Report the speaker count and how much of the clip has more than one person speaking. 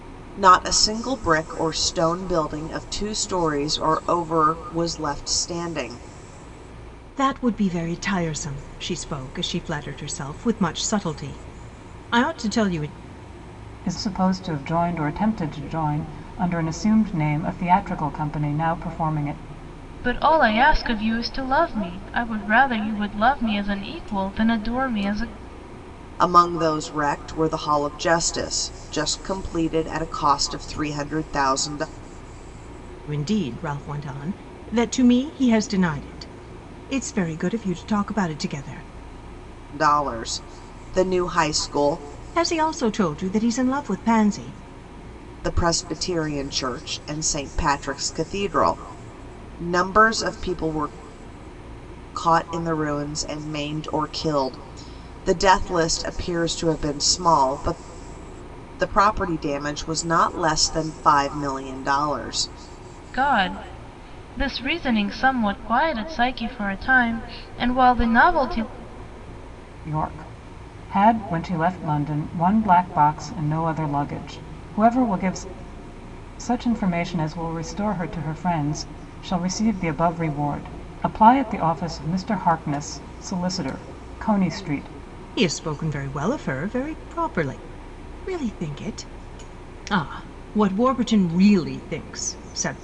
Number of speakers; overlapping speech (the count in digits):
4, no overlap